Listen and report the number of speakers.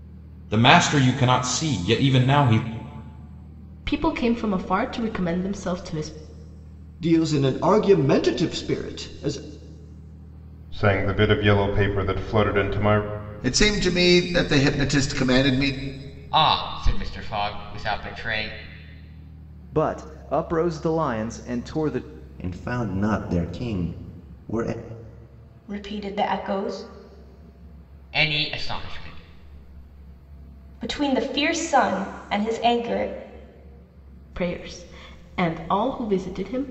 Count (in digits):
9